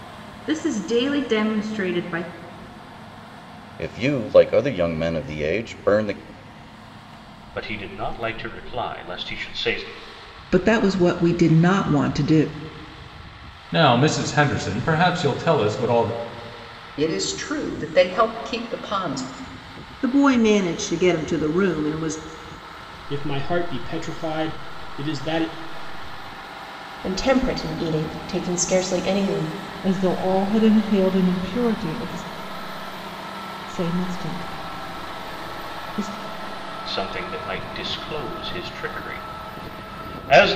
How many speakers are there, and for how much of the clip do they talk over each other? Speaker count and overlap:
10, no overlap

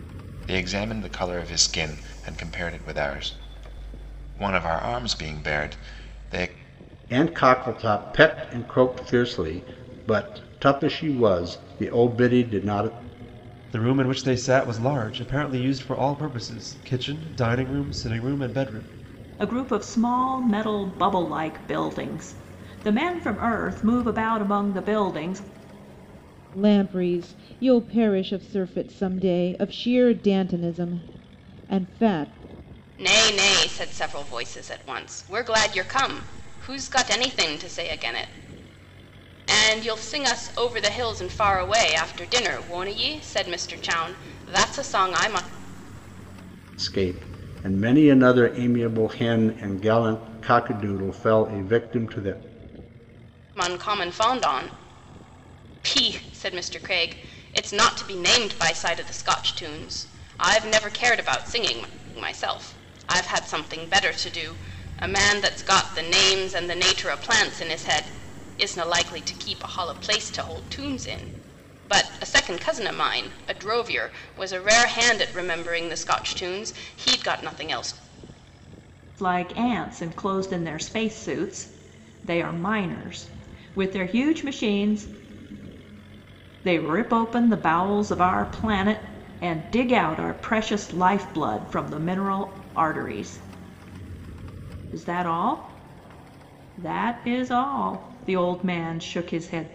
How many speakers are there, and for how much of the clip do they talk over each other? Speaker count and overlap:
6, no overlap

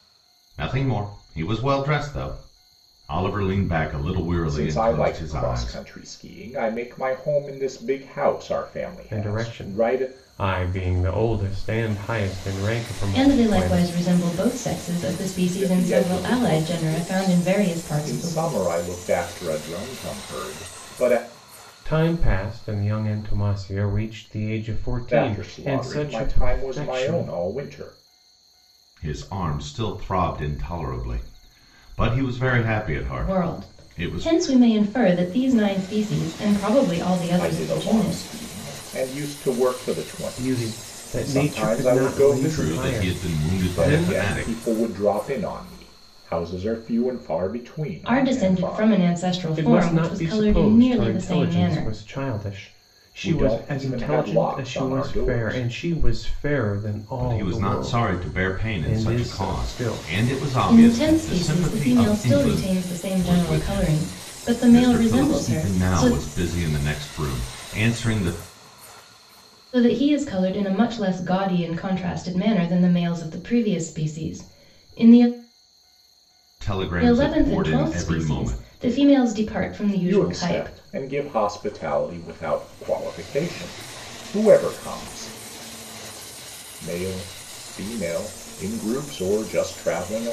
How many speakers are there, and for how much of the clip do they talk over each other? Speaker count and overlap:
4, about 34%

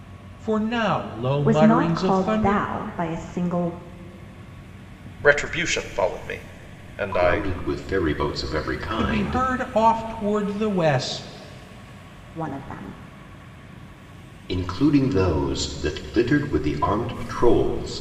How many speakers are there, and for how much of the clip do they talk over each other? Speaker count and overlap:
4, about 12%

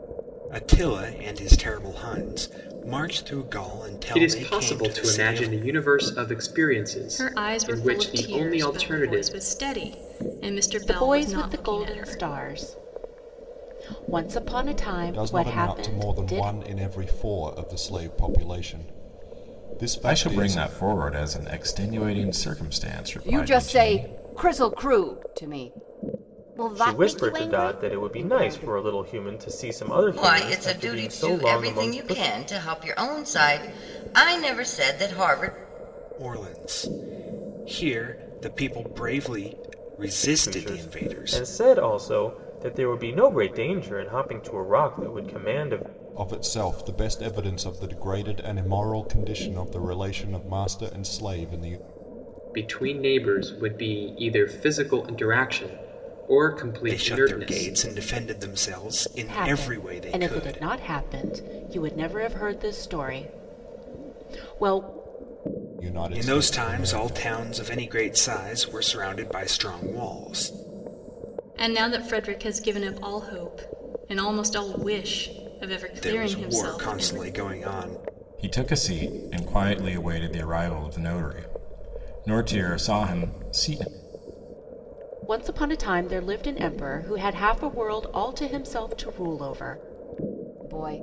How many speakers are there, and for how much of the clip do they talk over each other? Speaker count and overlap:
9, about 20%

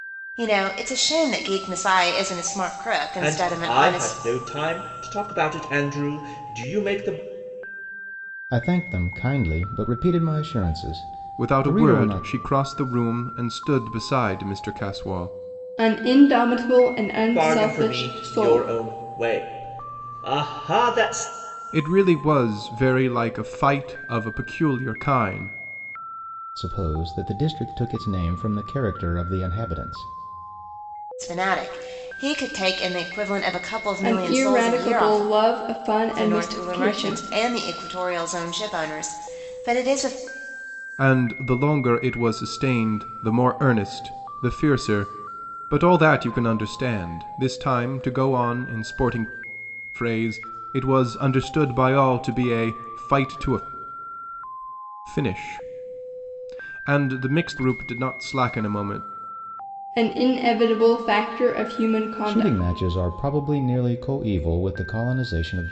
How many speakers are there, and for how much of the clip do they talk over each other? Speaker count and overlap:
5, about 10%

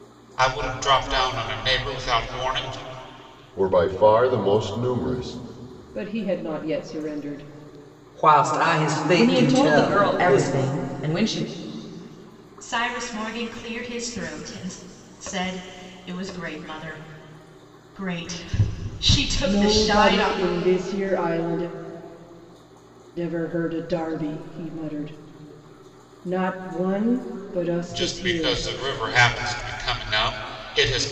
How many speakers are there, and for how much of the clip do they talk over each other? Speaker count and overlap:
6, about 10%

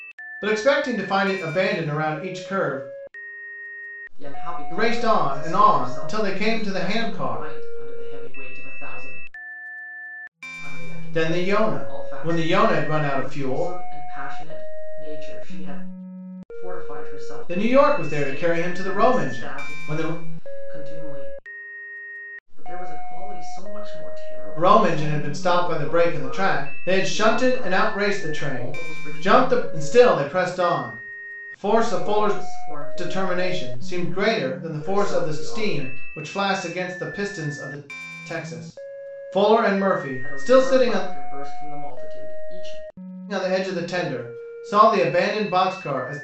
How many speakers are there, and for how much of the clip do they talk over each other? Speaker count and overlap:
2, about 39%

